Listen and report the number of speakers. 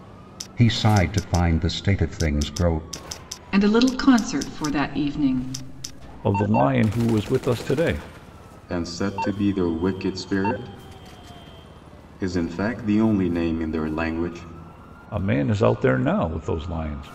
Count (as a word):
four